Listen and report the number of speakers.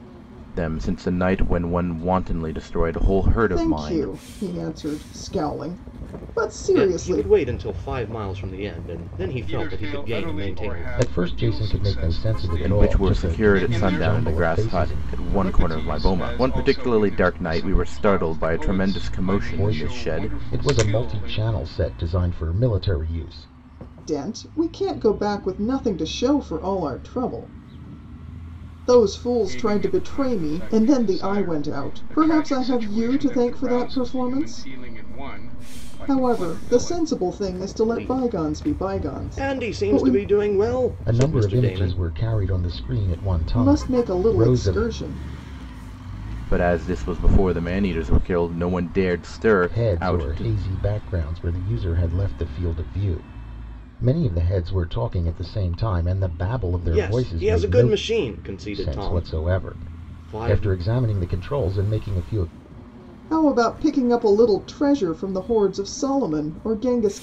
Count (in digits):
5